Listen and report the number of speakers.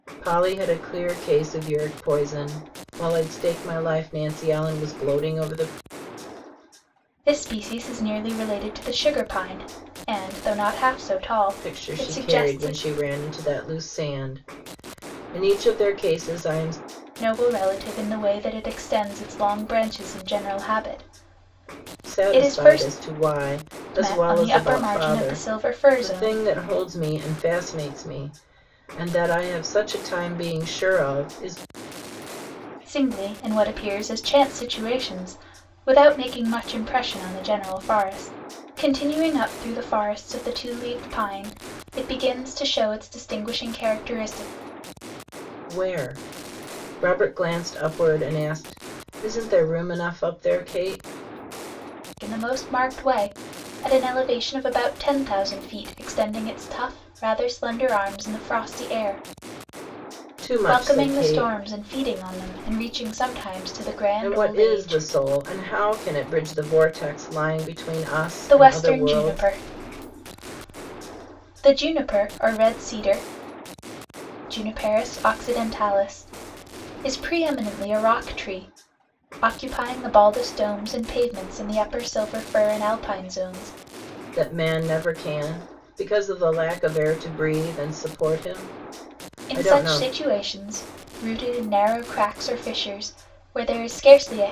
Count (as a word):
two